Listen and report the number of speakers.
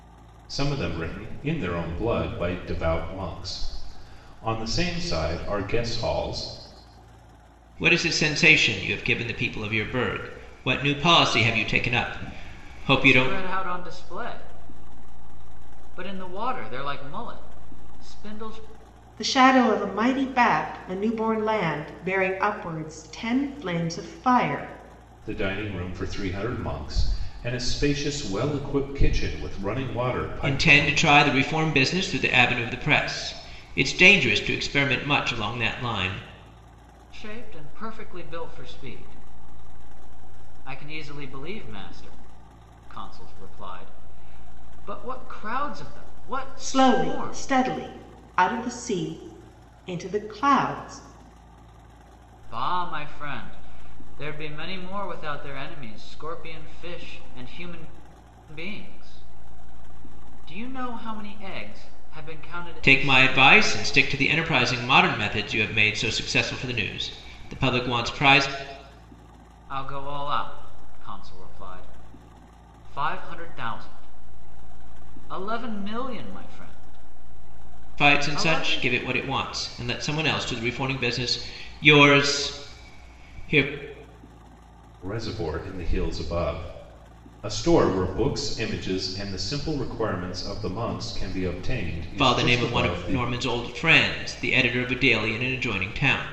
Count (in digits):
4